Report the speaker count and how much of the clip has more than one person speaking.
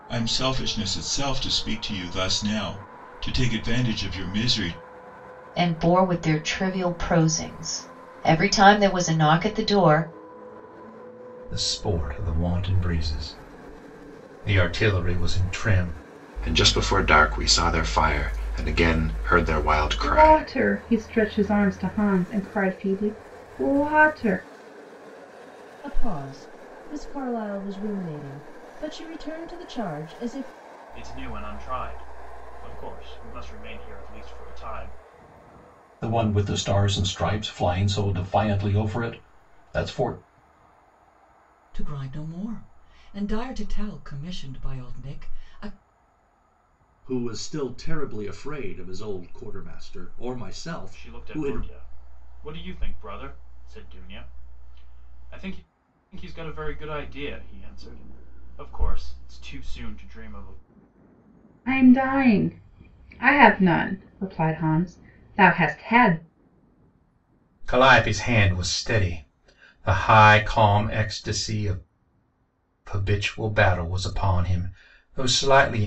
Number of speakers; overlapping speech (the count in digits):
10, about 1%